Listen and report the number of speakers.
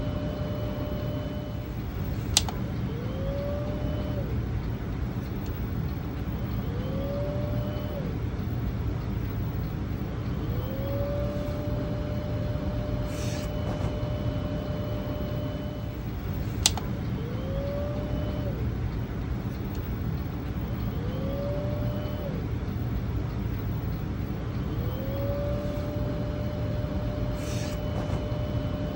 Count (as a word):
zero